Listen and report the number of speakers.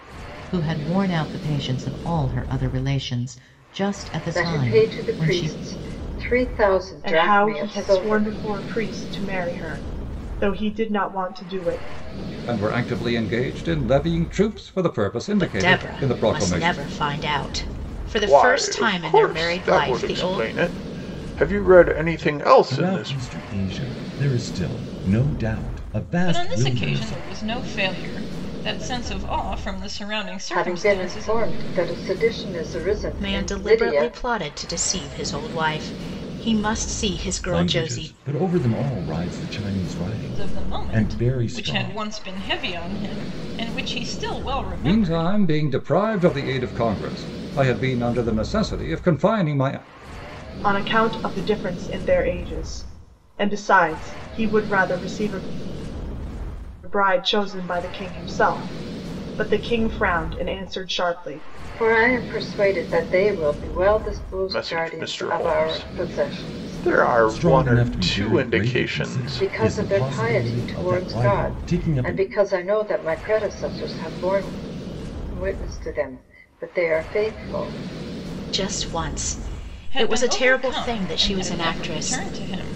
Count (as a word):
eight